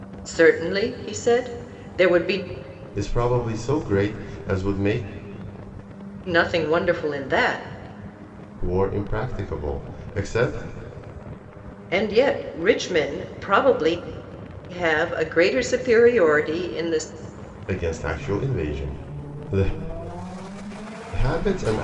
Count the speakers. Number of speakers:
2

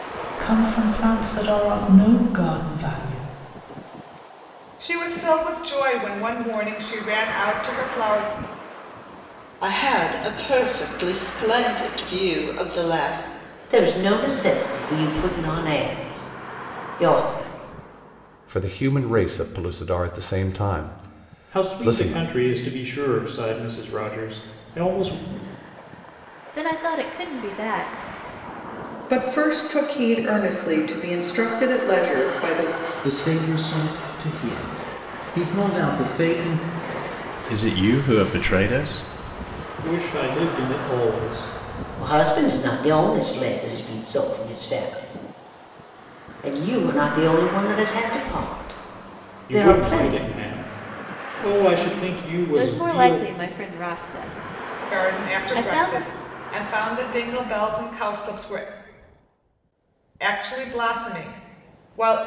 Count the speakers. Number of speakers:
10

